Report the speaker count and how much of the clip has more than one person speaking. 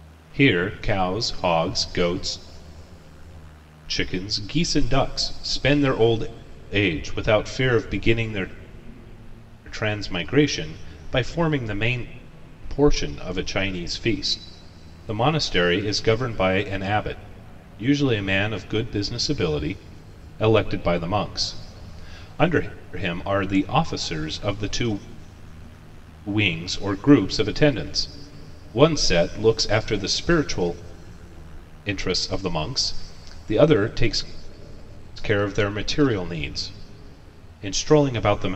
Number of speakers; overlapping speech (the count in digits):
1, no overlap